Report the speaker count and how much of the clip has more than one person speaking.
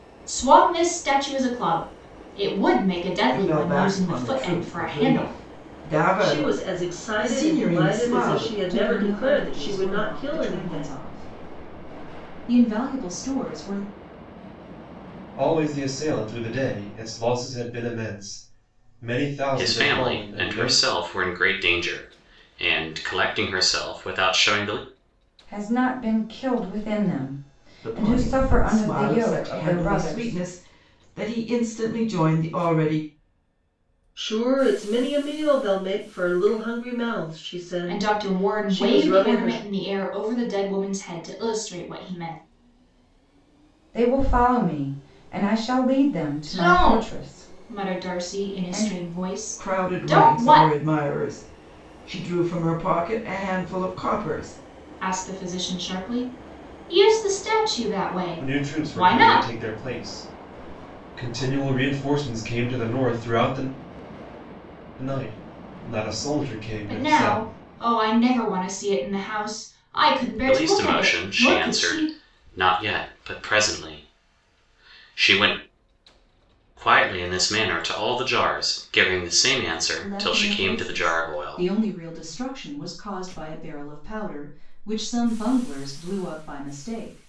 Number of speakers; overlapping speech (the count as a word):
seven, about 24%